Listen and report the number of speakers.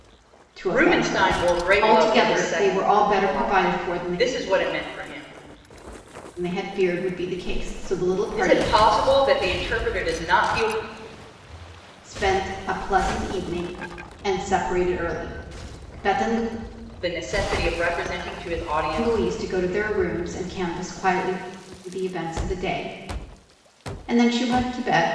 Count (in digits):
2